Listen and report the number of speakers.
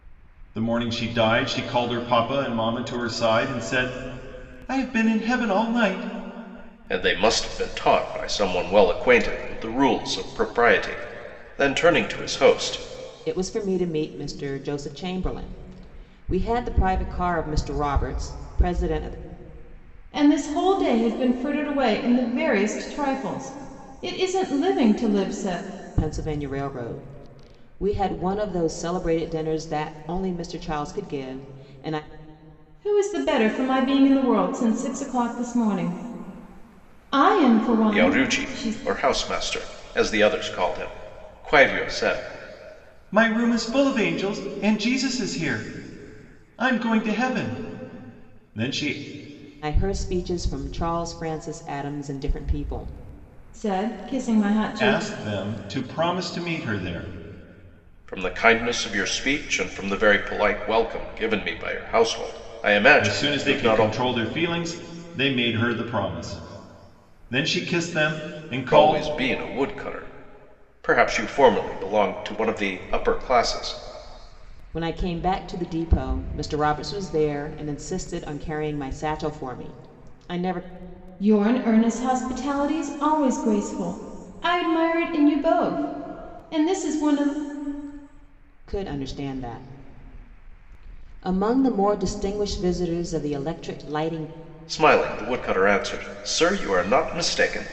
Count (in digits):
4